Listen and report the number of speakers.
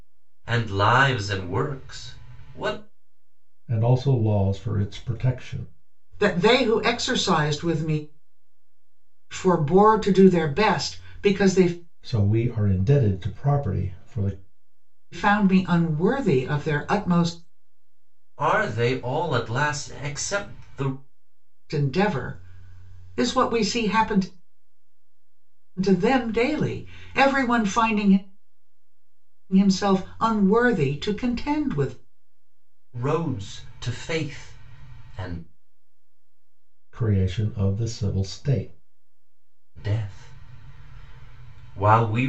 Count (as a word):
three